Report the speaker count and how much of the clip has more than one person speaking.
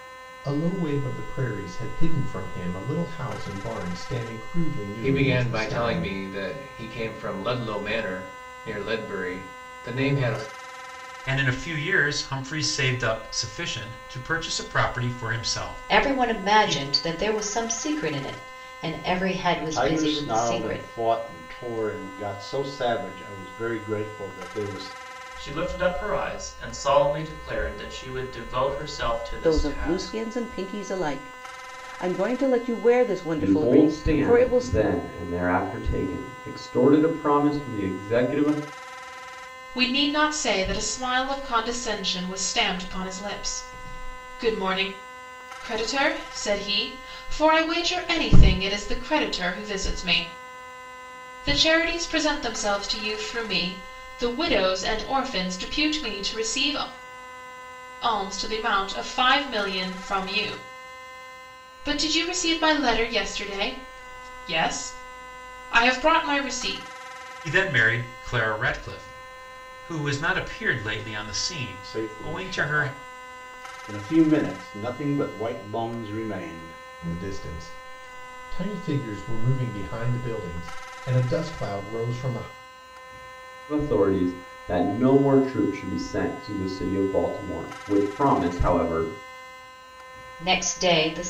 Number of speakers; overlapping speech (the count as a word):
nine, about 7%